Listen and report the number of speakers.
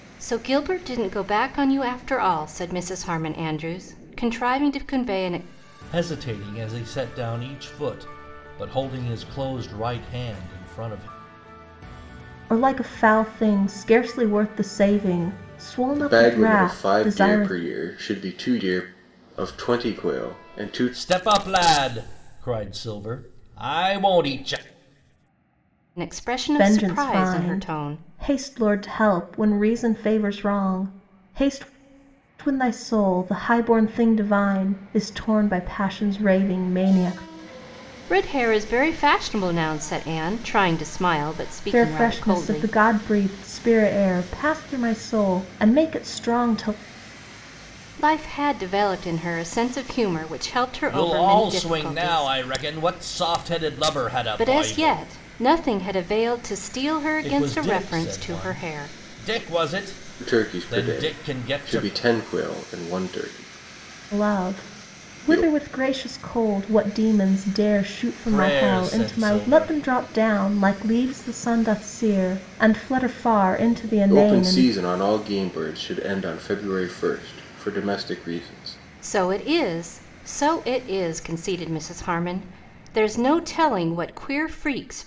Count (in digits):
4